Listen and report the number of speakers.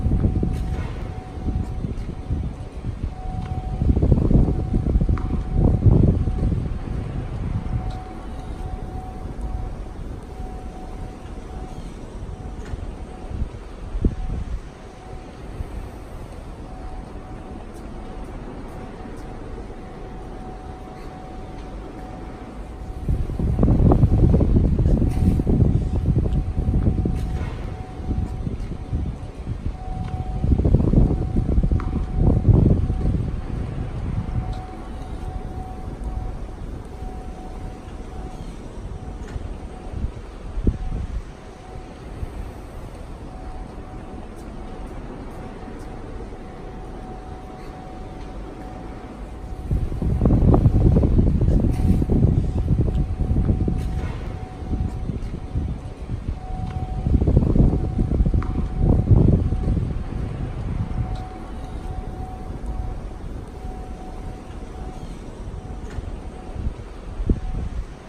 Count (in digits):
0